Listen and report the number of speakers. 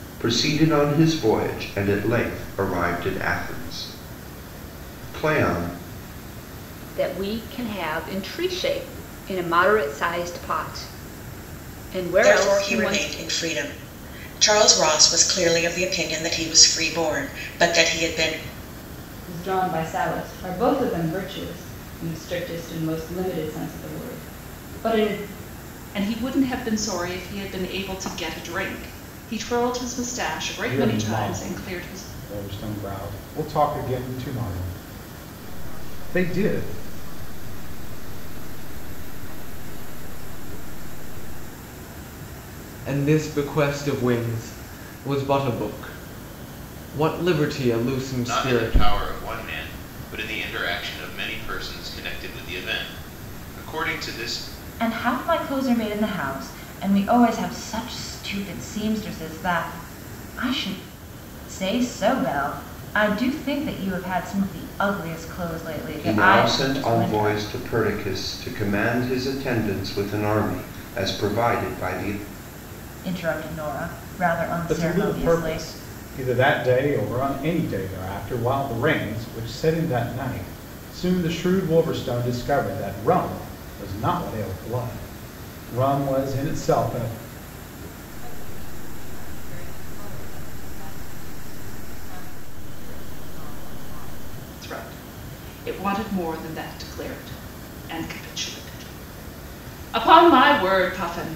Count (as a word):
ten